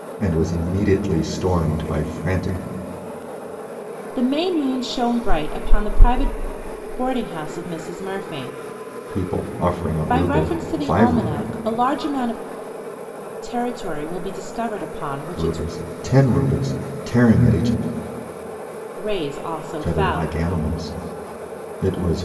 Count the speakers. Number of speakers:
2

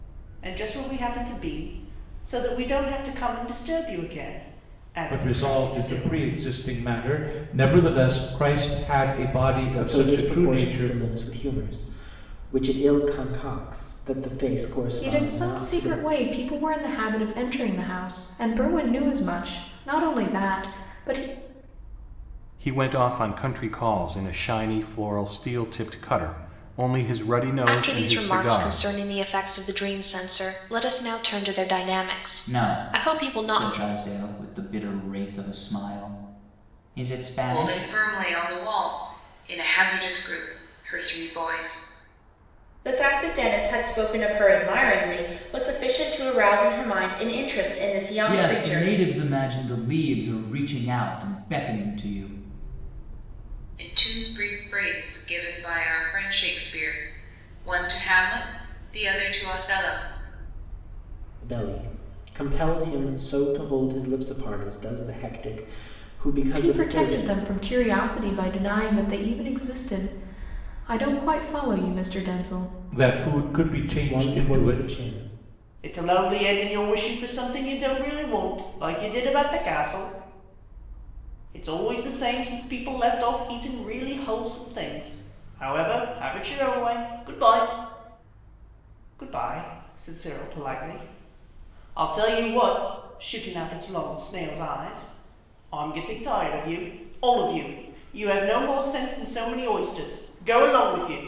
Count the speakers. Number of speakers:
9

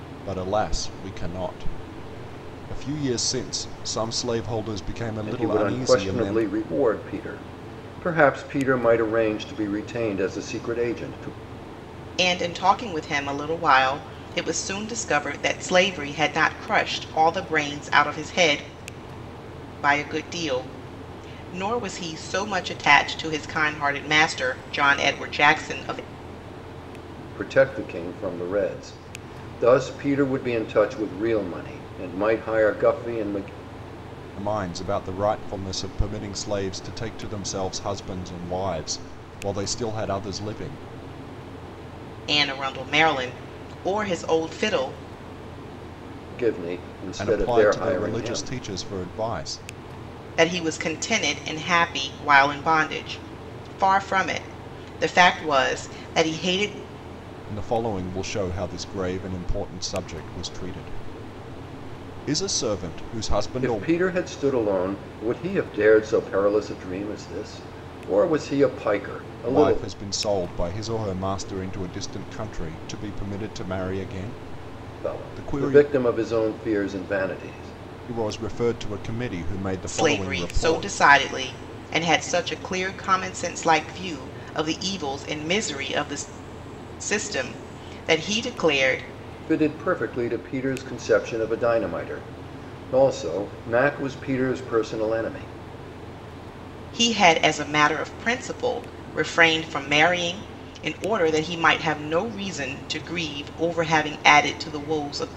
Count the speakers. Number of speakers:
3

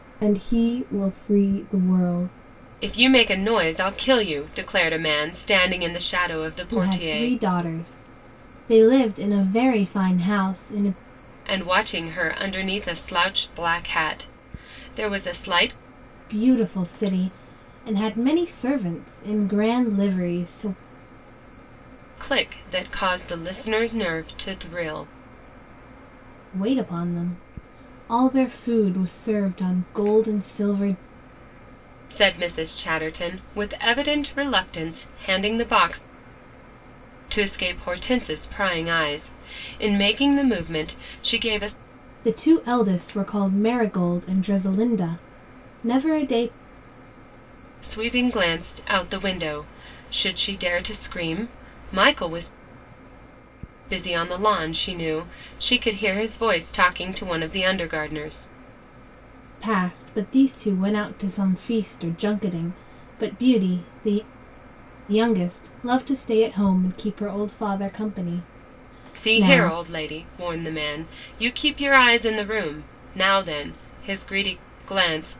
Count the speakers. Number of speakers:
2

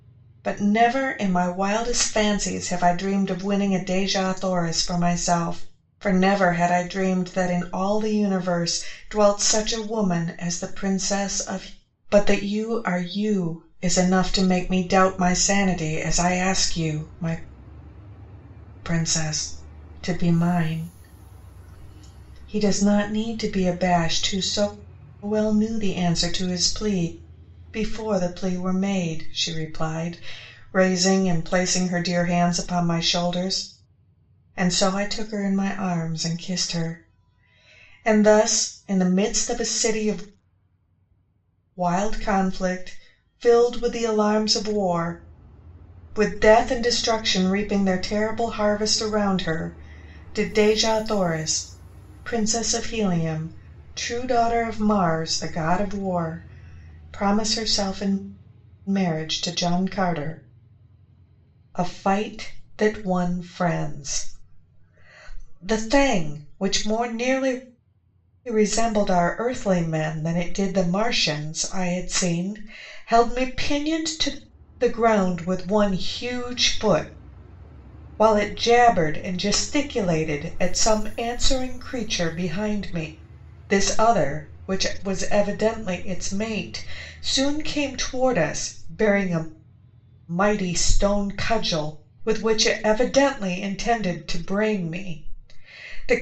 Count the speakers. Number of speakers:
1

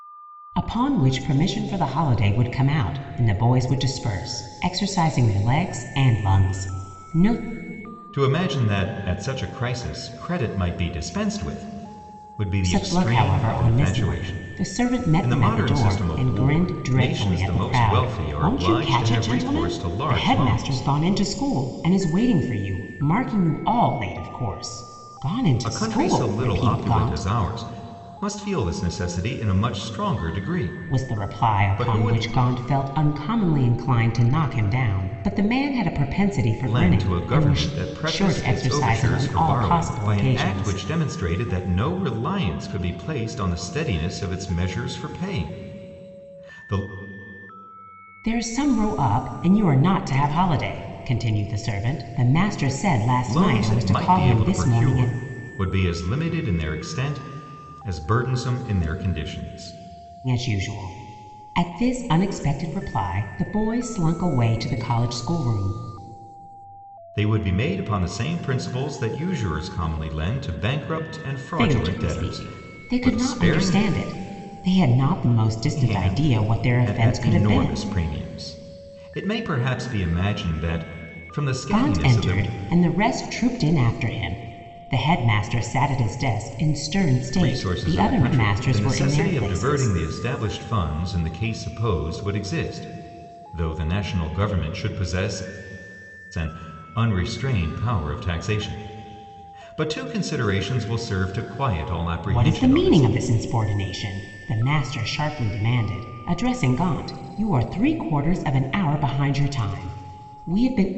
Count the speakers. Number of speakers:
2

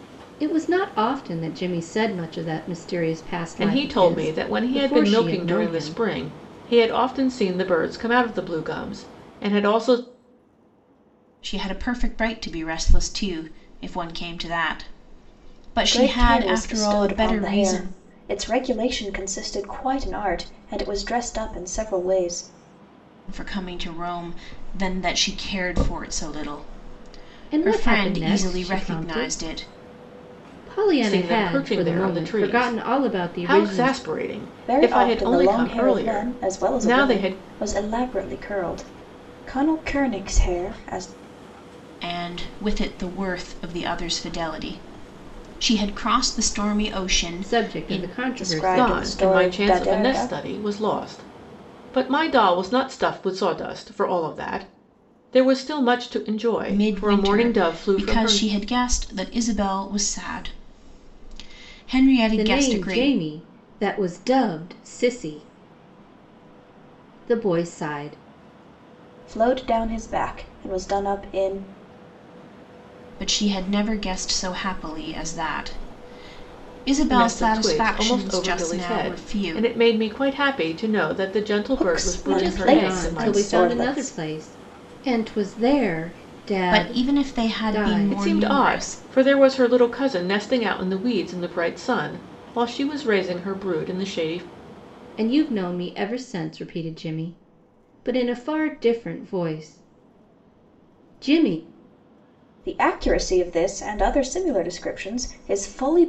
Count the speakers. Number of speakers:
4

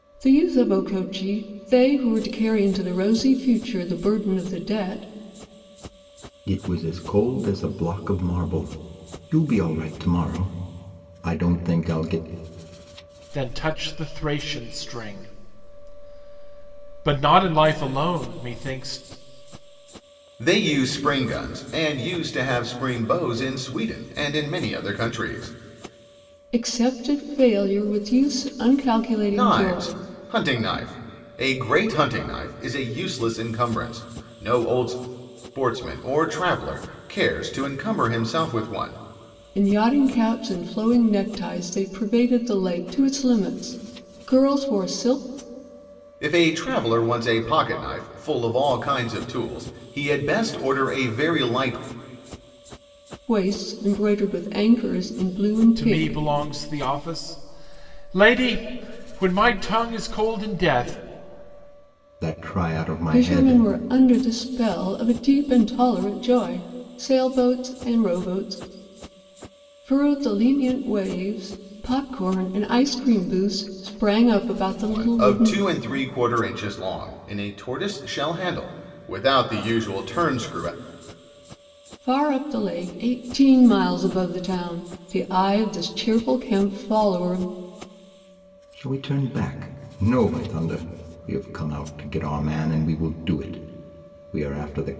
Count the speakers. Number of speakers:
4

